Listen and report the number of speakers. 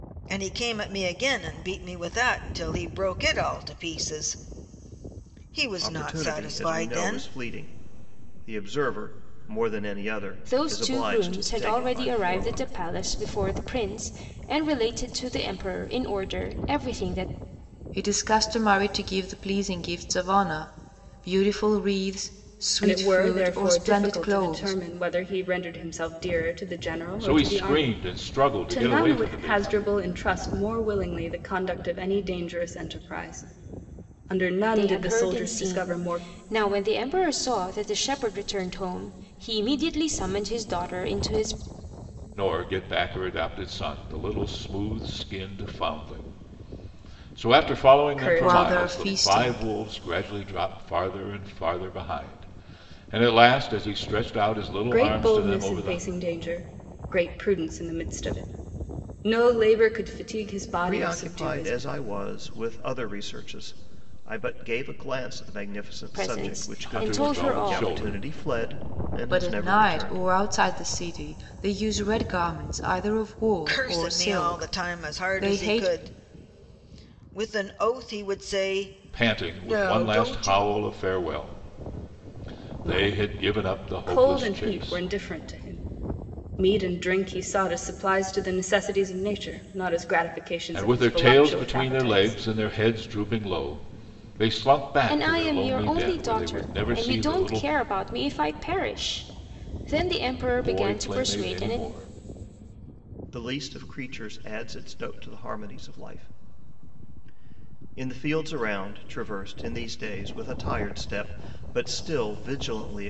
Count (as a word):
six